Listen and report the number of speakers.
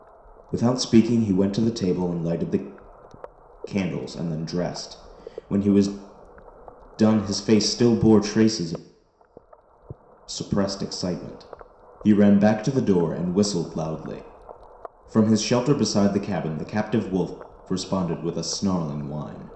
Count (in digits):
1